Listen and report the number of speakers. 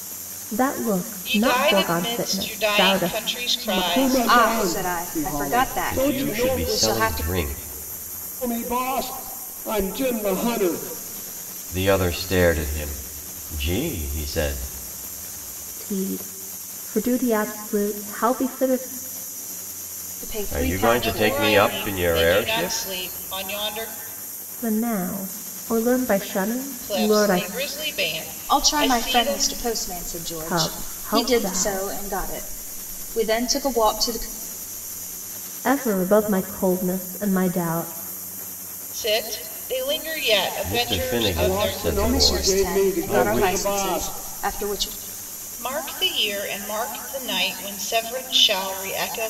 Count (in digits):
5